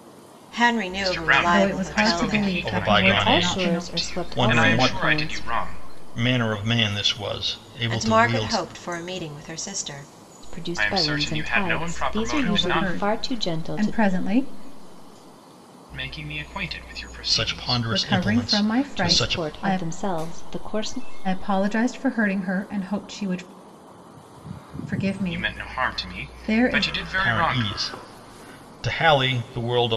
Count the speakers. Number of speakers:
5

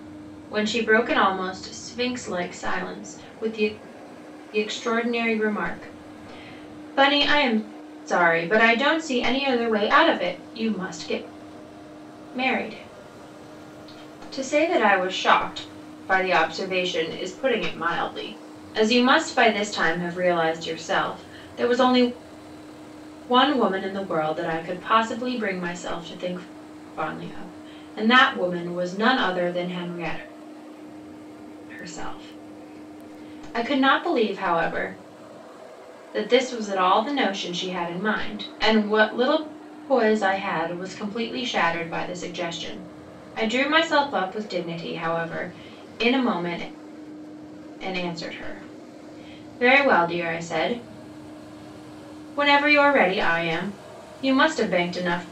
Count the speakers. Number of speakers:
1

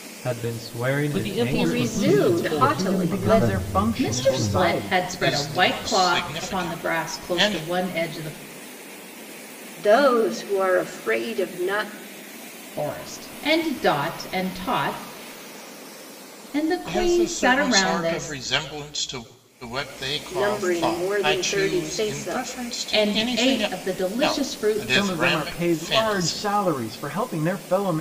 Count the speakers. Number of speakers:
7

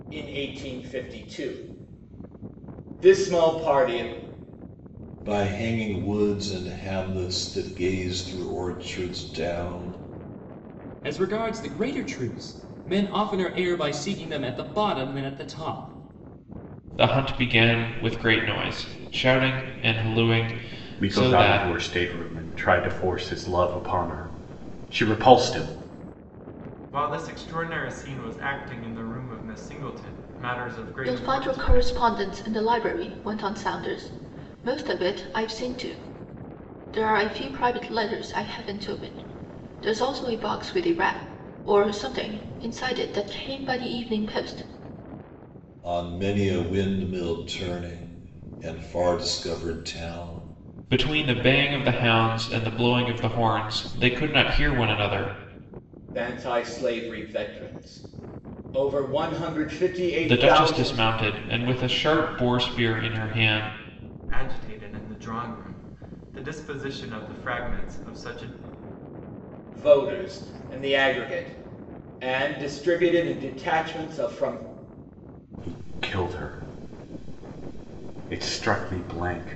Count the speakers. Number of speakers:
7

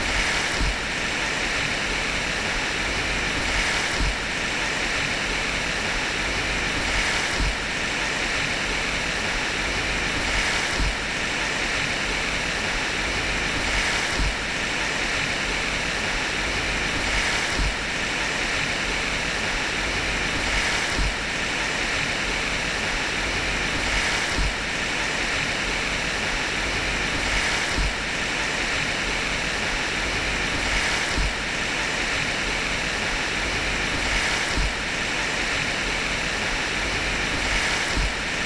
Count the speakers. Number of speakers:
0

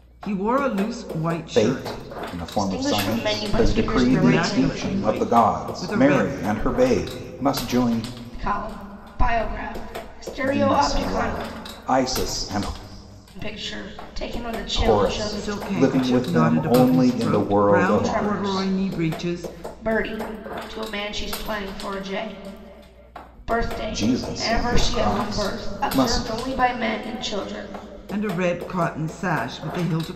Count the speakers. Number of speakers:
3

